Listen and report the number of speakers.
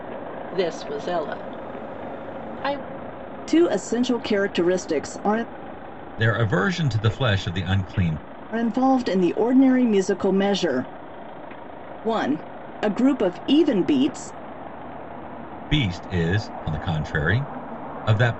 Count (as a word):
three